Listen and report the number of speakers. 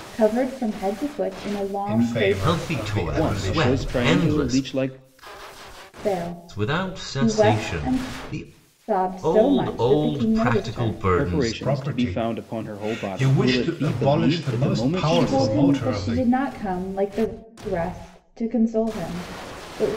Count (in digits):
4